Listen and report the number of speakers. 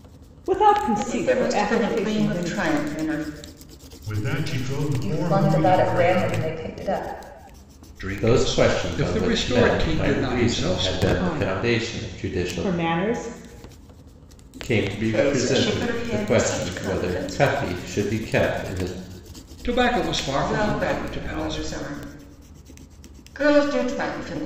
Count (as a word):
six